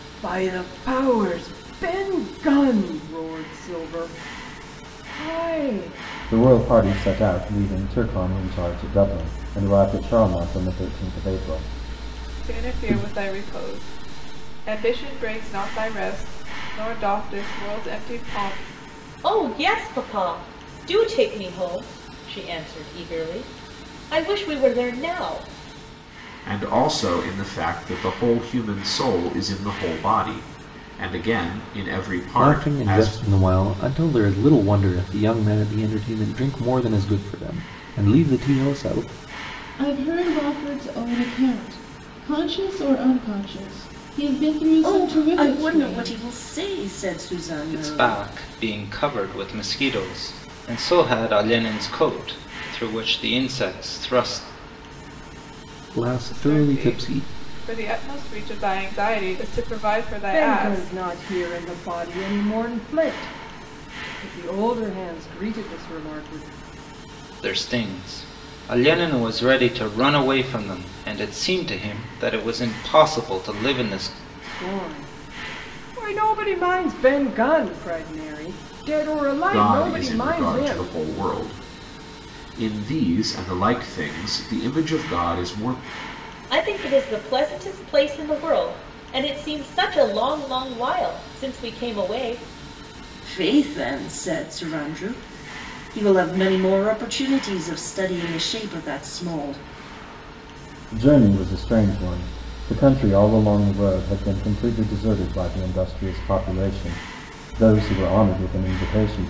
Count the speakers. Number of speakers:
nine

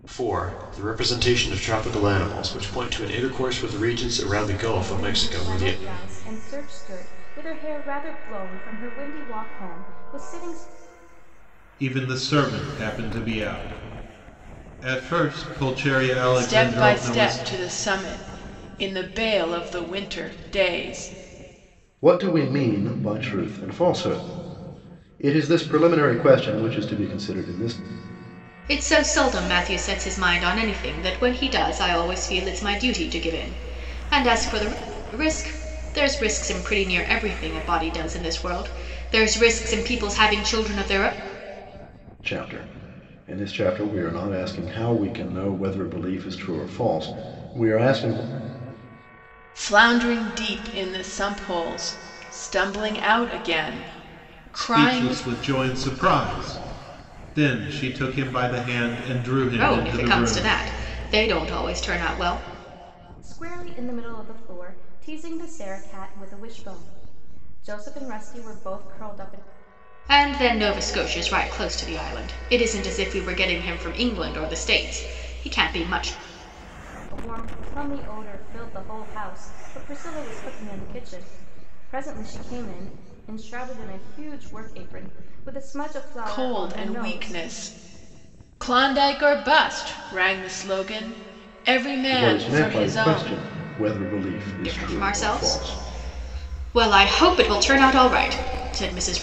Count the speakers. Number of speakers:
six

